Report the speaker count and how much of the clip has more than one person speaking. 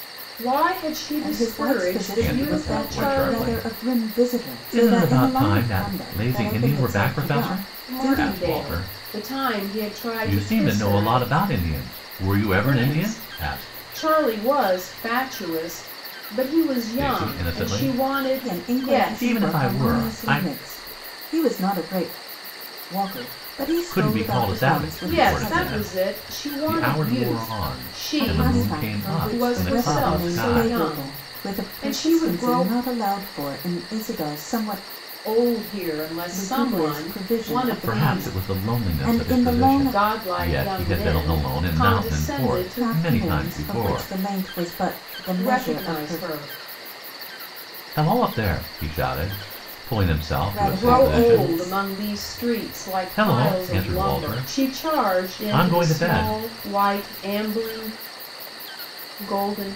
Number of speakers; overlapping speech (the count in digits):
3, about 59%